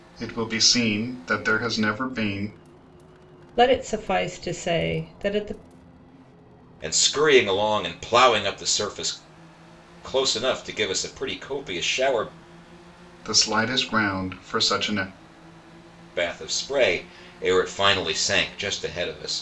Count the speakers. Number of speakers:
three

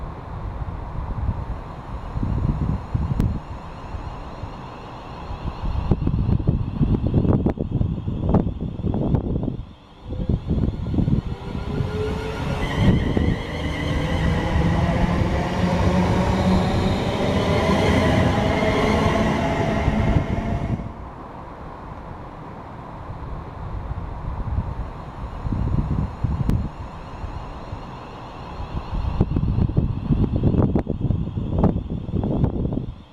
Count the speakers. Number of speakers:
zero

